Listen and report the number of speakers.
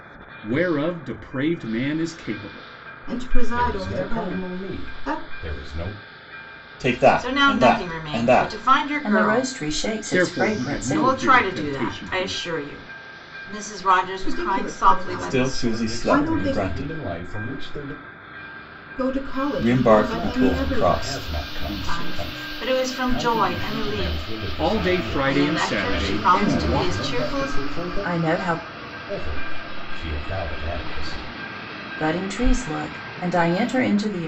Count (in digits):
6